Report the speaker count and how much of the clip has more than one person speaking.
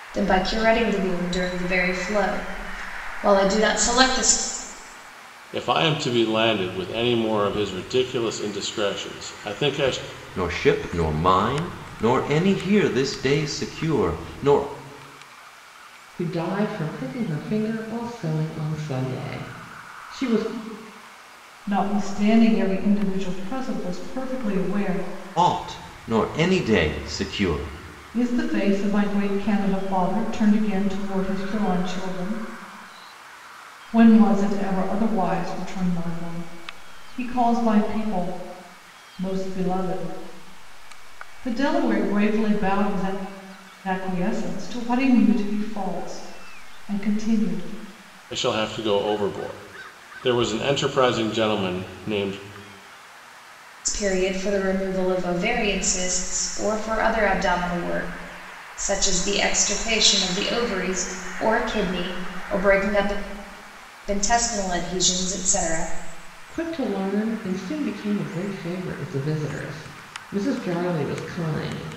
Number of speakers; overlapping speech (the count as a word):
five, no overlap